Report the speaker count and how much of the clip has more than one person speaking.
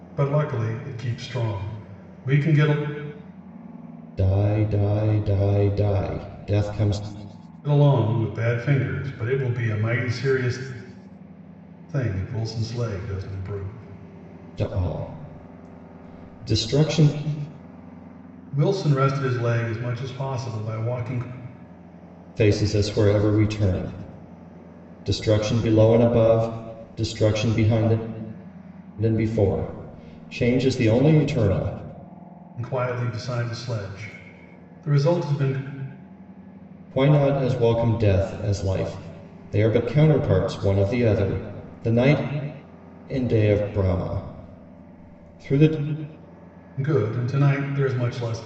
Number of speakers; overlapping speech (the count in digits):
2, no overlap